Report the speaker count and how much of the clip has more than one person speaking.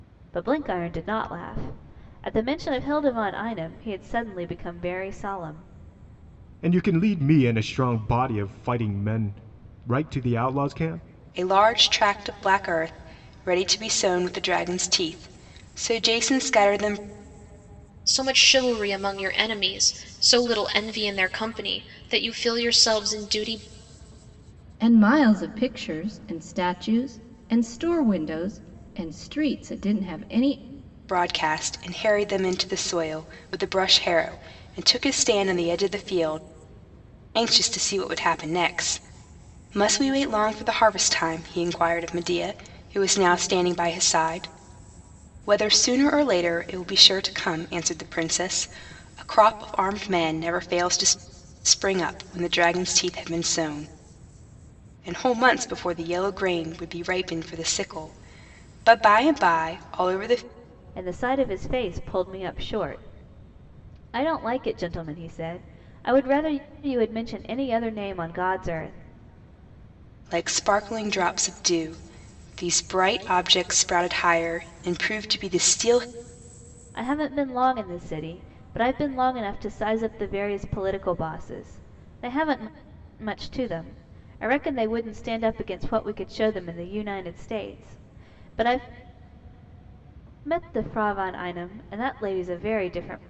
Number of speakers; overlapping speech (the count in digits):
5, no overlap